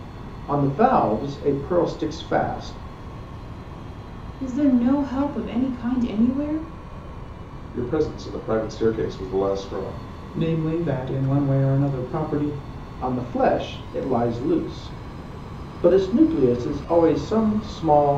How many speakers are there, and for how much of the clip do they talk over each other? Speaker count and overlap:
4, no overlap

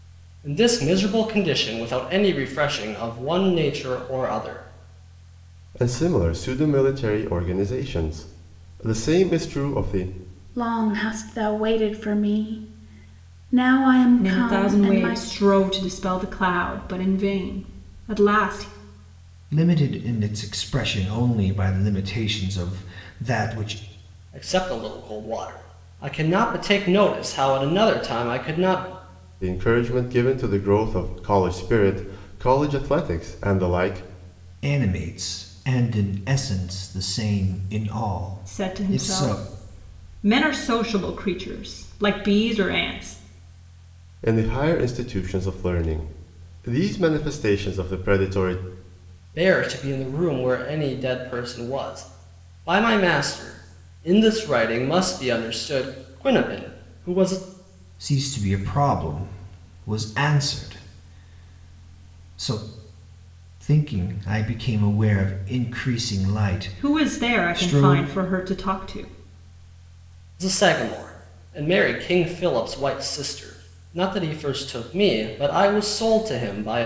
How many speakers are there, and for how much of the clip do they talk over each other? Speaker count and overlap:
5, about 4%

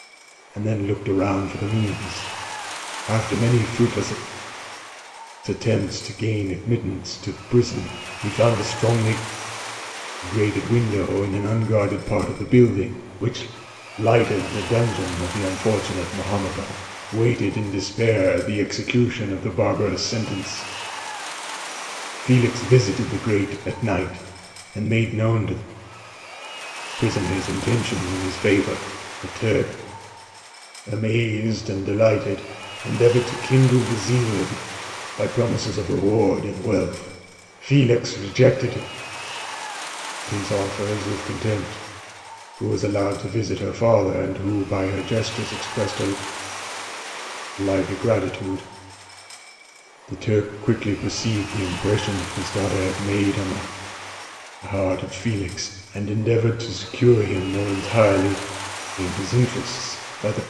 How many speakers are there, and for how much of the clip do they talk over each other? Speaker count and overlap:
1, no overlap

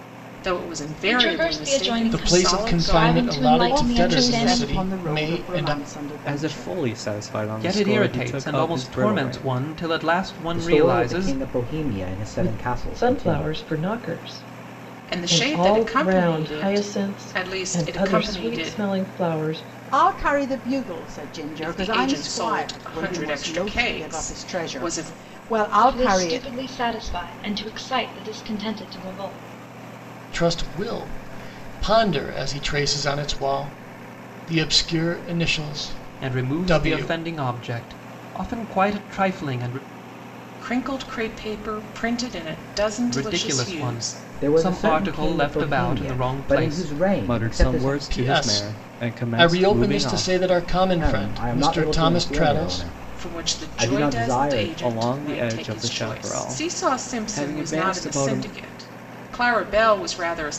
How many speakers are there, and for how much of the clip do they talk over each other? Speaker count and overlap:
8, about 53%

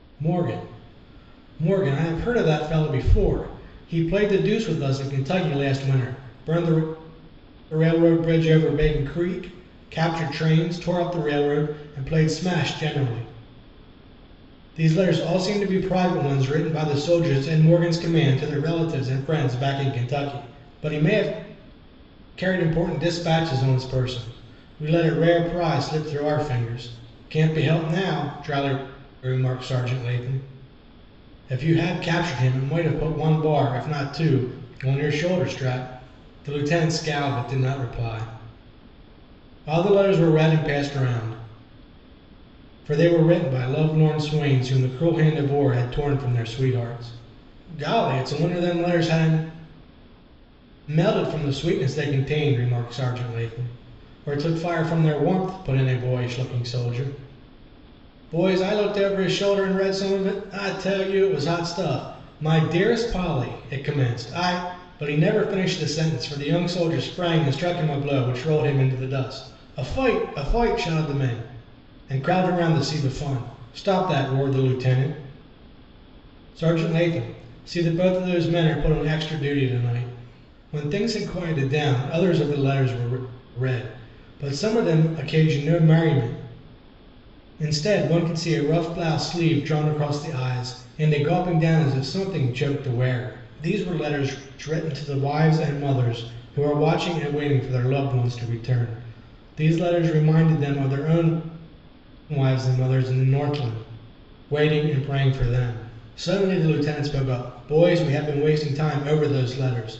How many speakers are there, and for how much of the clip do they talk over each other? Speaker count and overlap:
1, no overlap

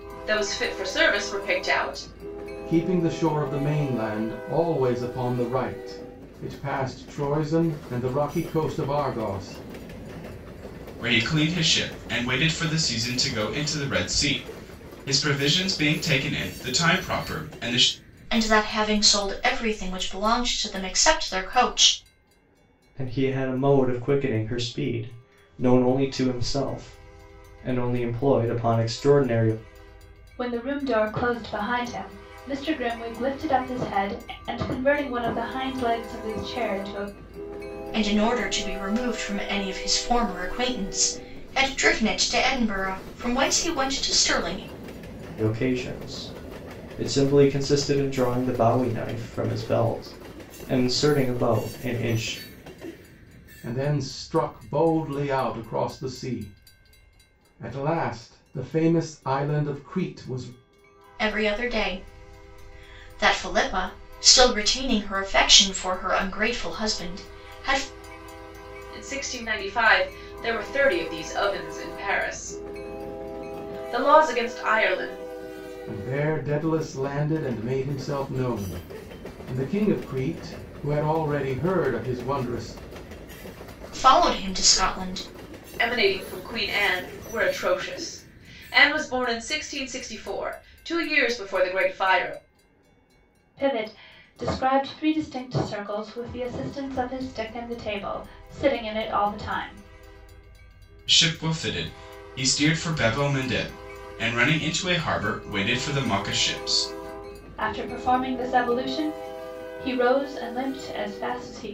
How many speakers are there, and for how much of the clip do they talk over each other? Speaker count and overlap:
6, no overlap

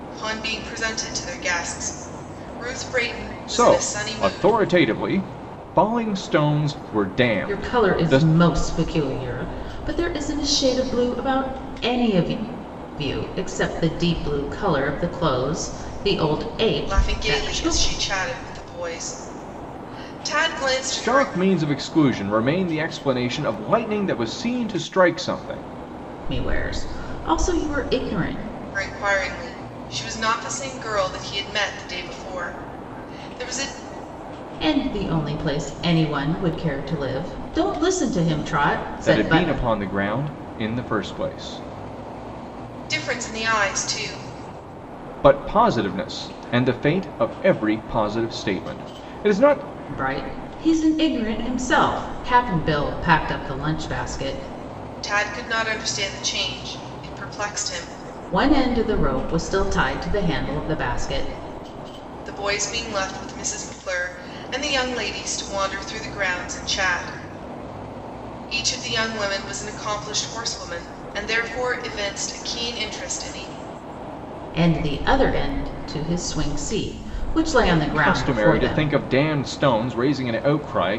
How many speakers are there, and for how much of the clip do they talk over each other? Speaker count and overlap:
3, about 6%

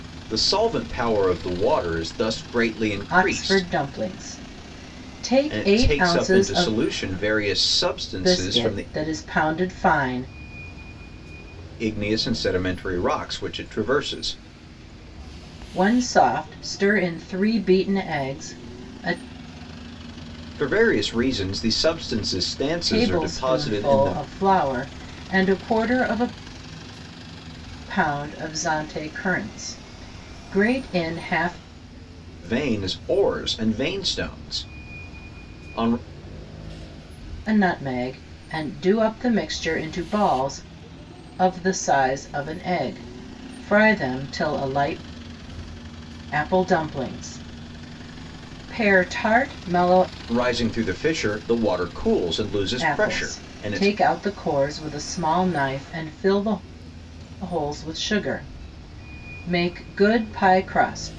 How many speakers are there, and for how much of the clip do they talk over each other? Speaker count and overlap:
2, about 9%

